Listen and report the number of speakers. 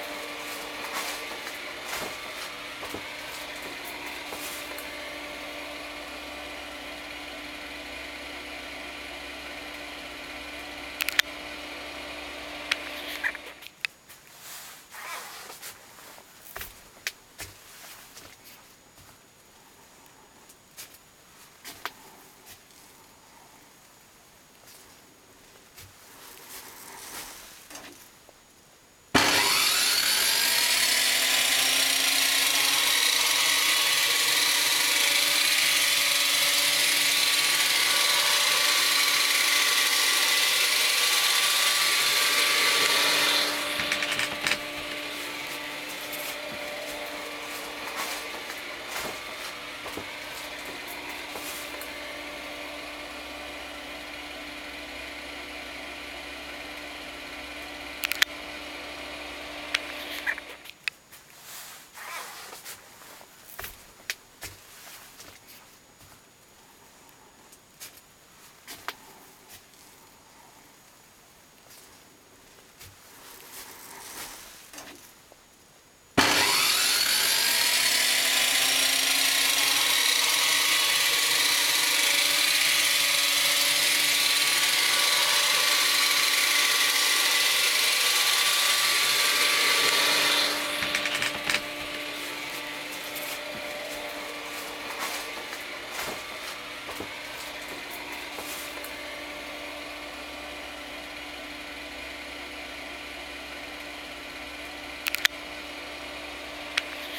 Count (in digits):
0